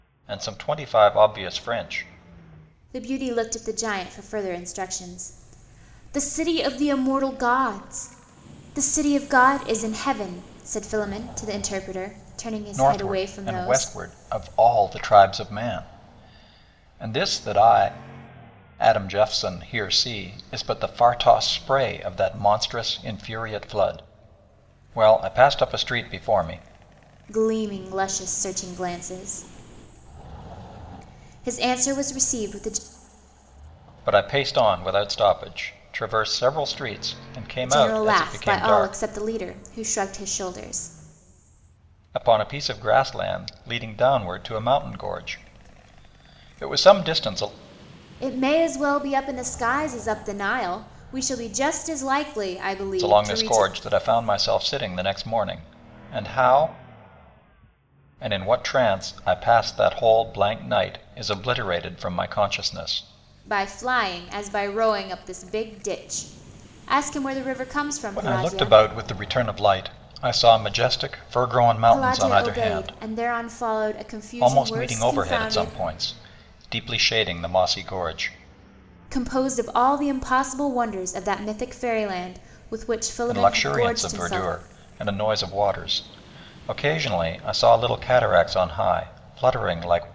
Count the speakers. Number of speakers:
2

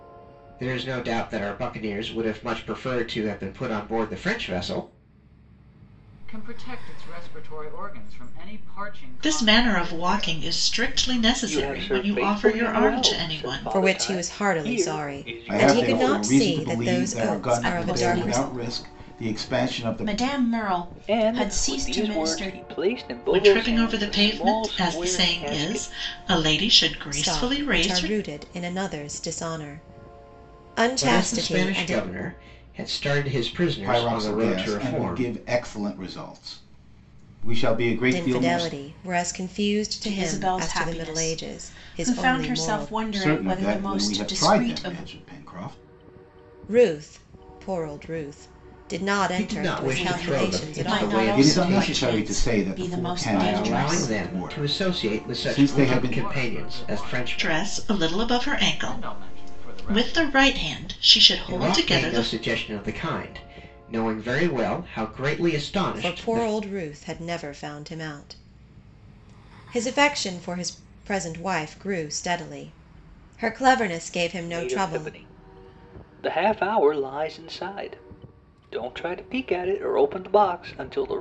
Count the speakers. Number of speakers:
7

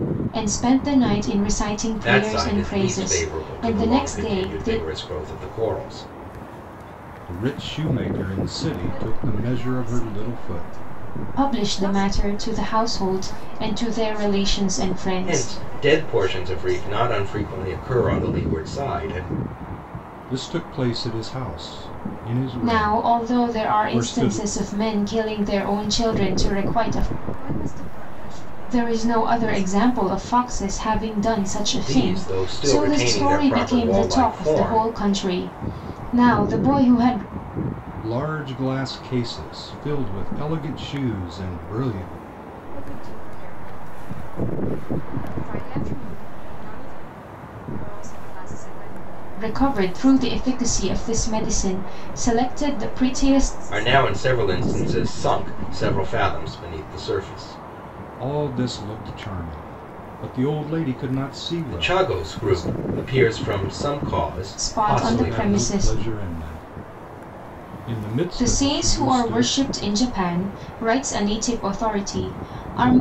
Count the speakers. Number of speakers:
4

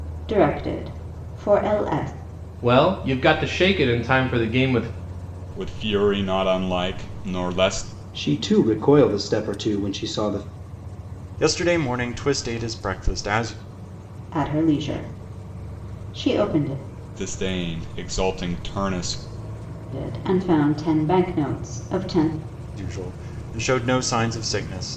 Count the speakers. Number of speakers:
5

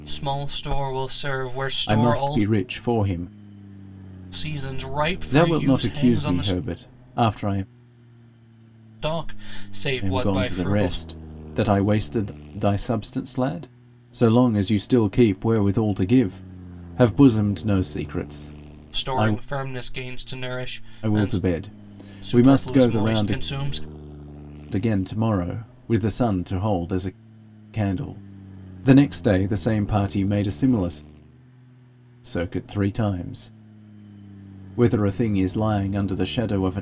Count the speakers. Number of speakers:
2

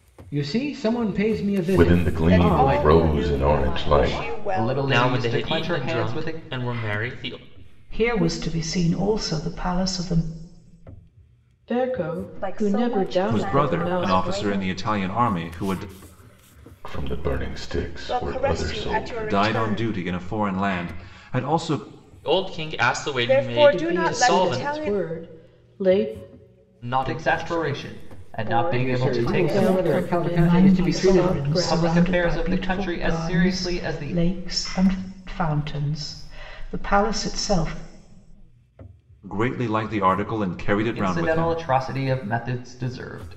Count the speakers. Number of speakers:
10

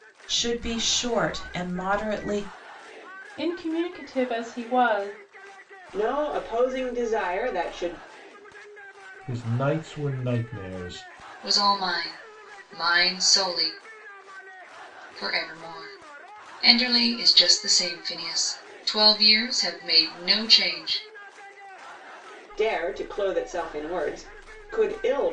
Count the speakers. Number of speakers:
5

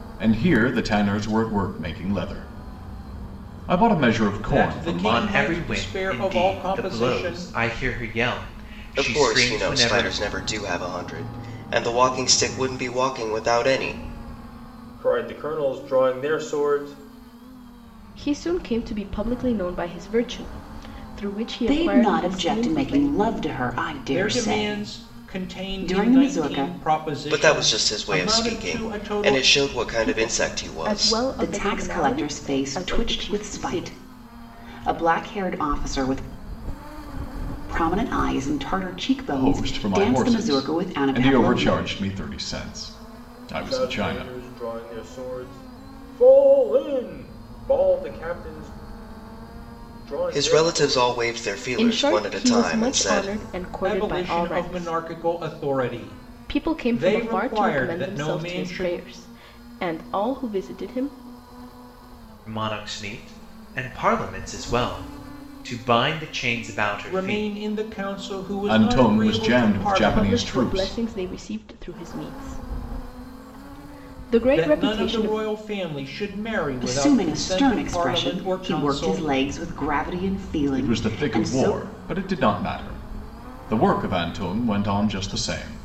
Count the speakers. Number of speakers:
7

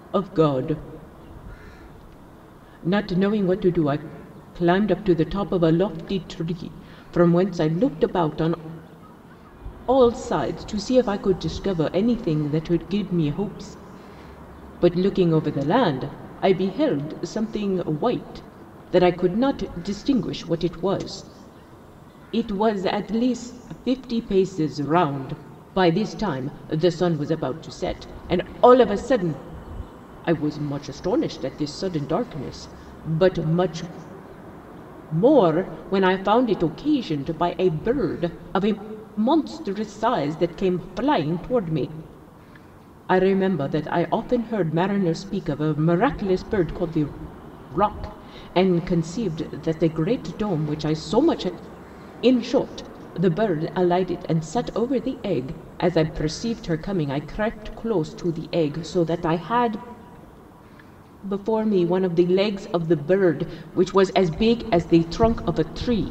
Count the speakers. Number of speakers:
1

